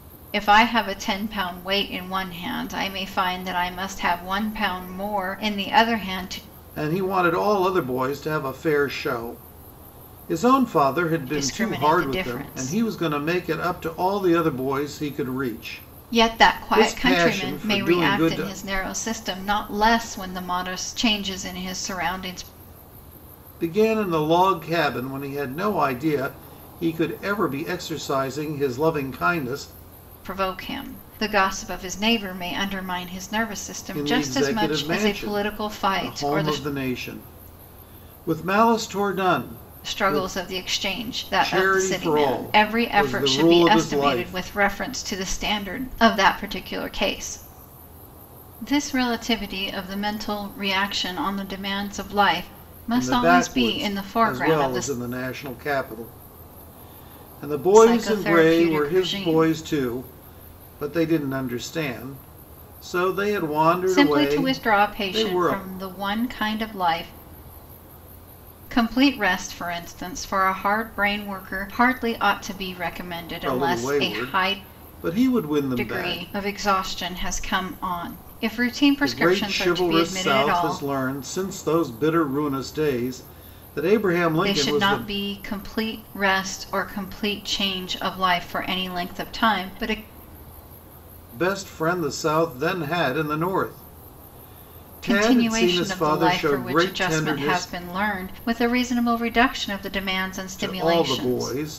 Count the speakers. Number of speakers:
2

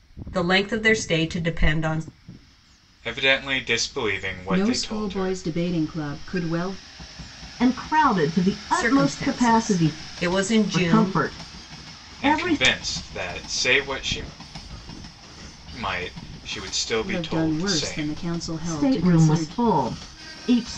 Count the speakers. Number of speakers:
4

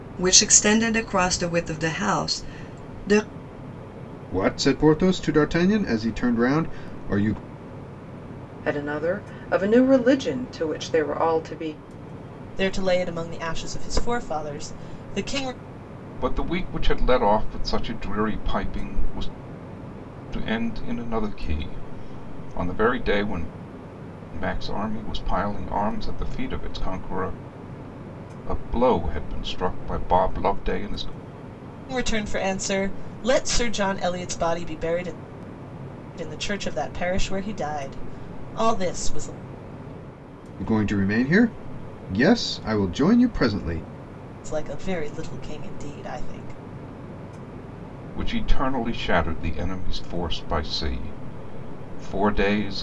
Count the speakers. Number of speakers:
5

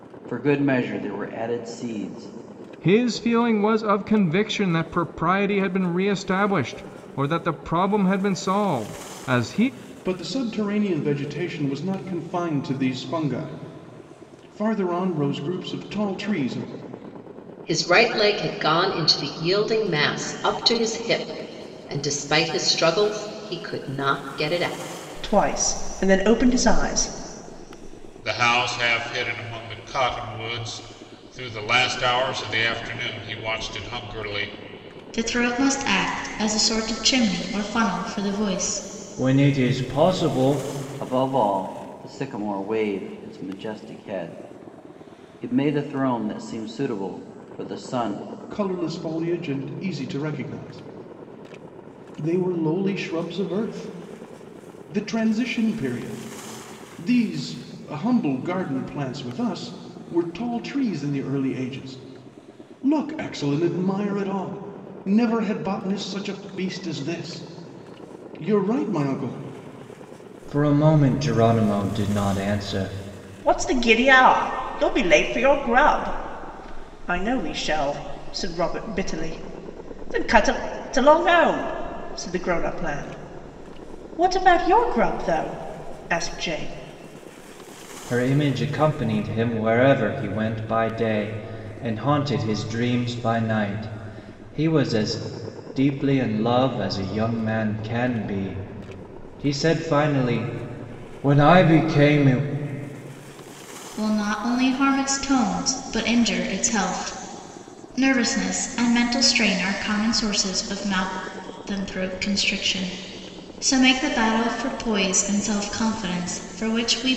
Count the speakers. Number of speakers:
8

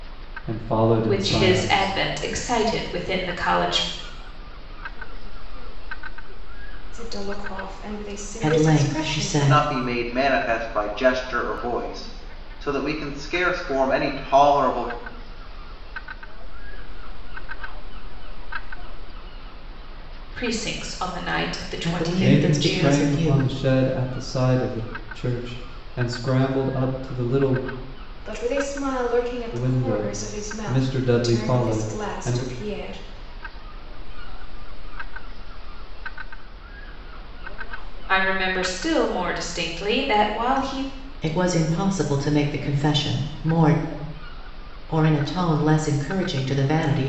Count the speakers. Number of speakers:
6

